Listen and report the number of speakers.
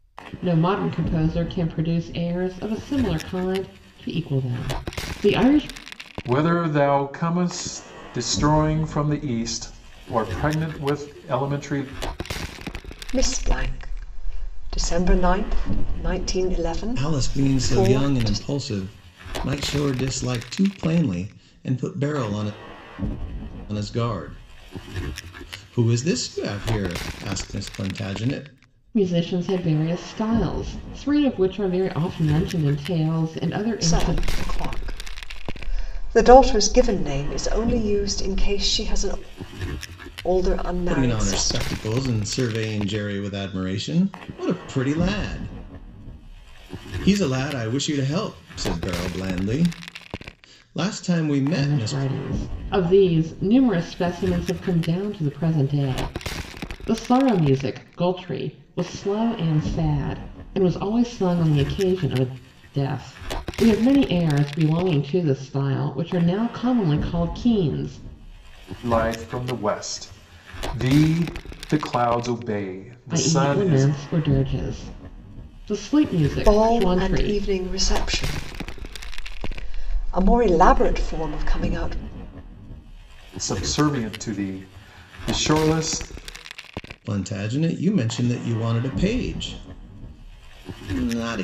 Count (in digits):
4